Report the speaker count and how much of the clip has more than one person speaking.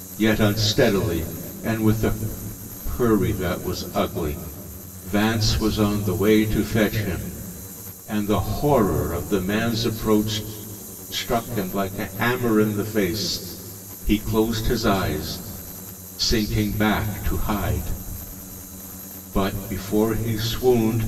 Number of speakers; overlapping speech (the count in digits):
1, no overlap